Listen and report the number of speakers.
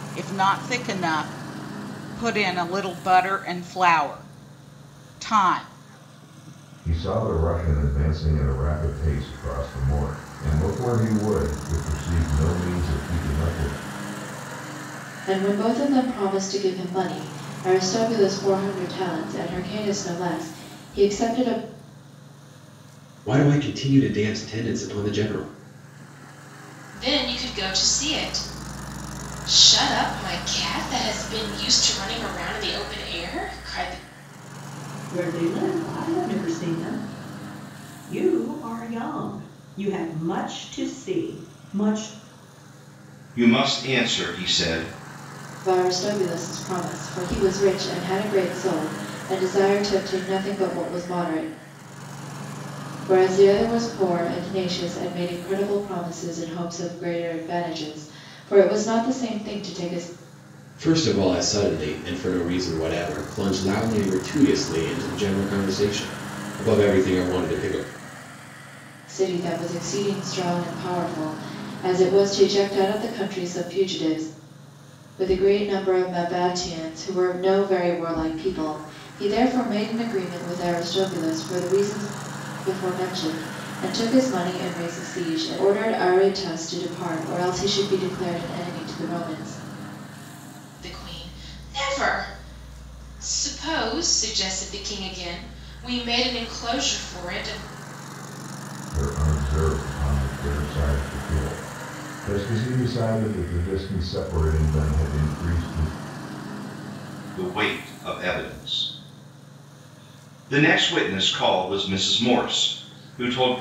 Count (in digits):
7